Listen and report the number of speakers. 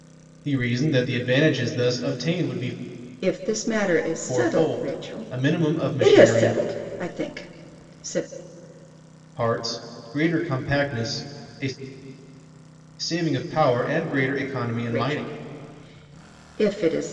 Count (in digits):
2